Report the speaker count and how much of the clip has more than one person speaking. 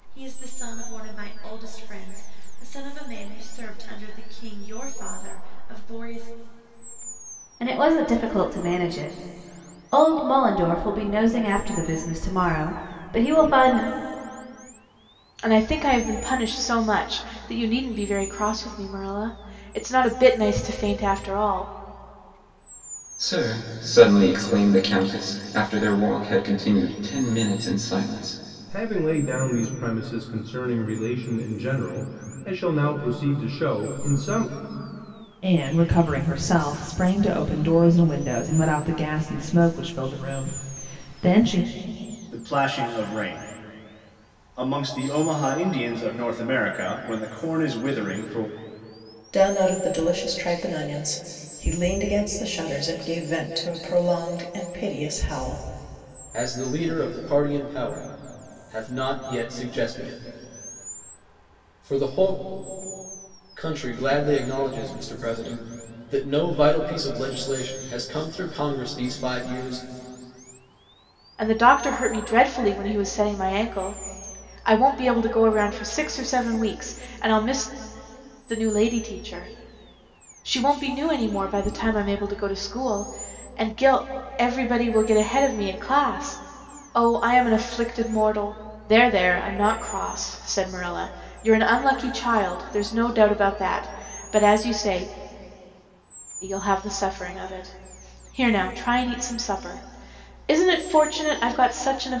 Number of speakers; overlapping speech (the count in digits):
9, no overlap